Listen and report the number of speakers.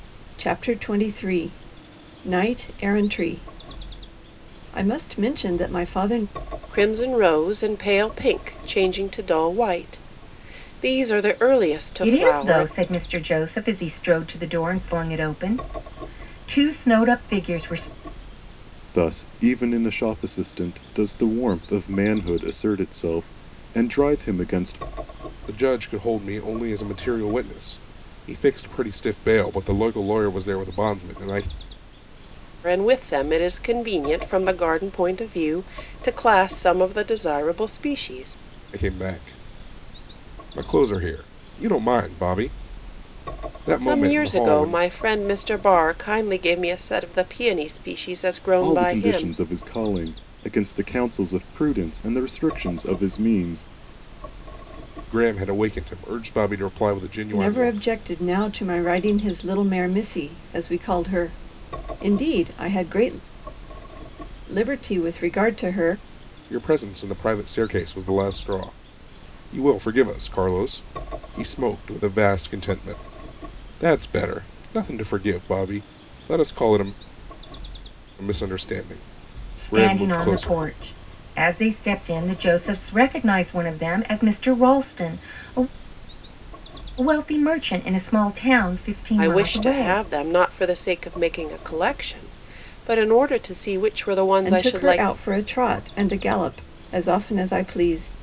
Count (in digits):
5